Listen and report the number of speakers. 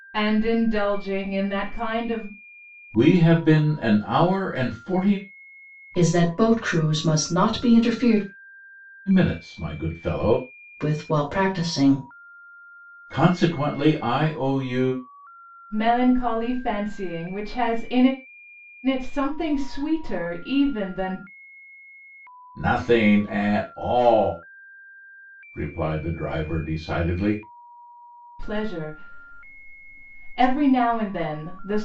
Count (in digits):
3